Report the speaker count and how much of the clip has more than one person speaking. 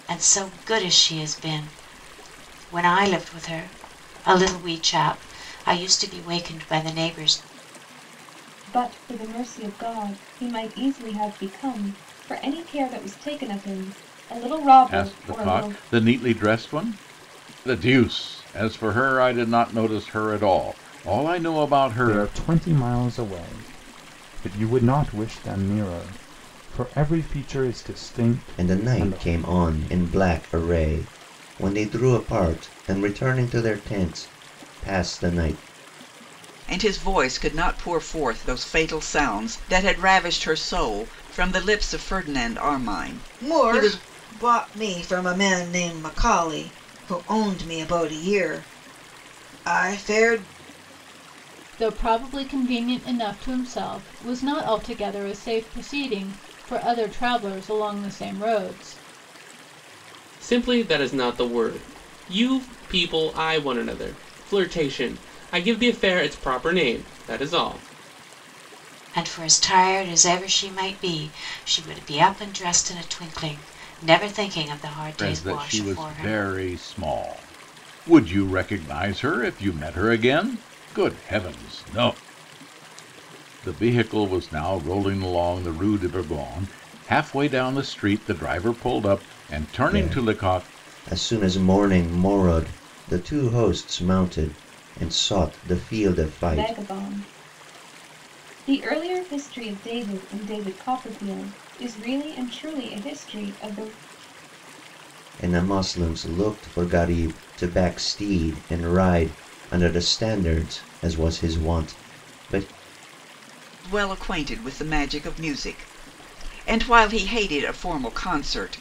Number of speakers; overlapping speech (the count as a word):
nine, about 4%